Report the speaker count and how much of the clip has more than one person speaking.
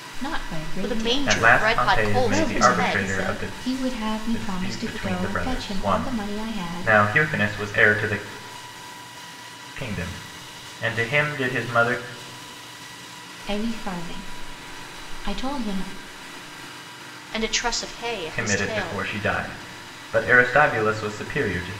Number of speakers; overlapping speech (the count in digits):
3, about 28%